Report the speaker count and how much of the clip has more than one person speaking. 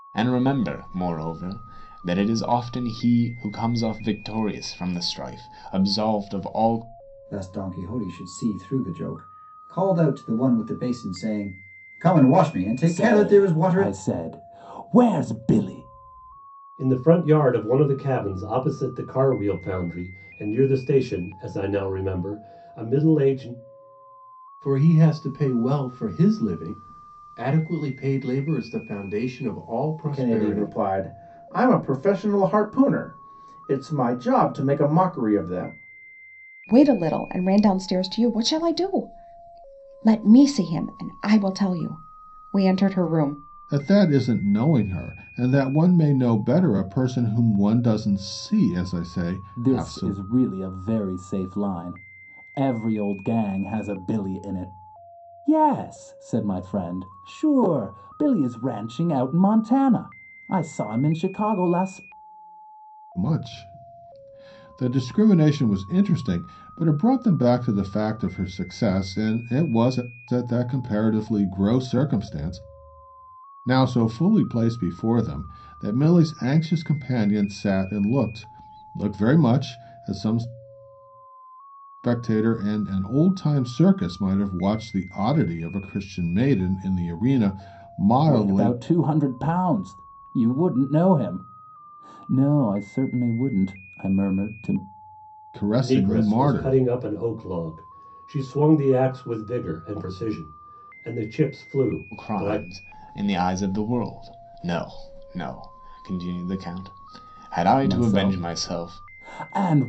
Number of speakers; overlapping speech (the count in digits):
8, about 5%